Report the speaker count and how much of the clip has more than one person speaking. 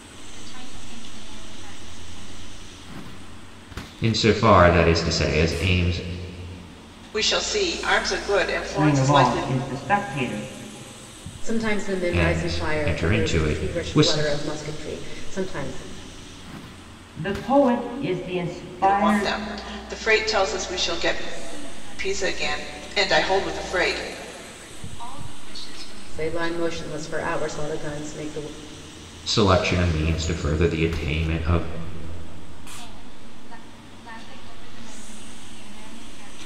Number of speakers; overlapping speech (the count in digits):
5, about 15%